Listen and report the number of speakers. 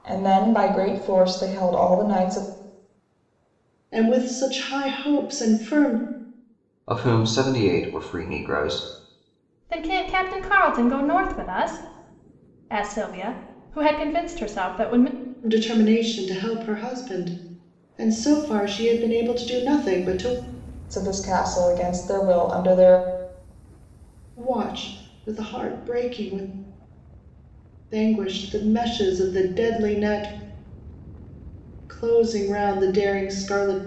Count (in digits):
4